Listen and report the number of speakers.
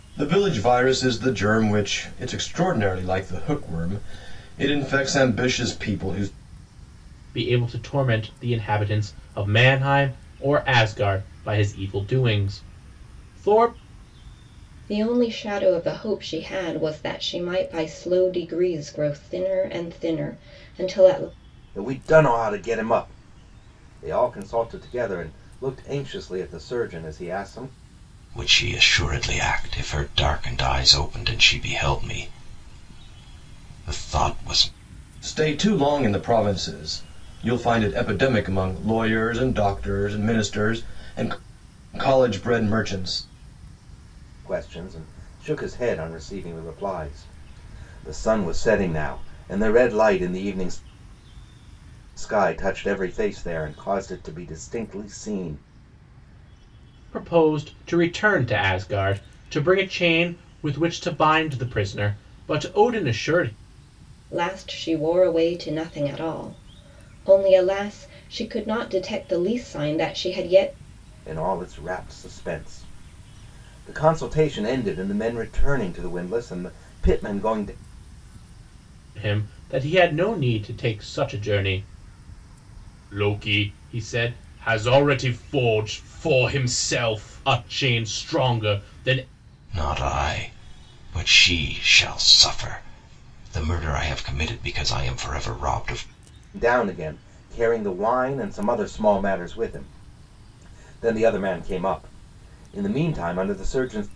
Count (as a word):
five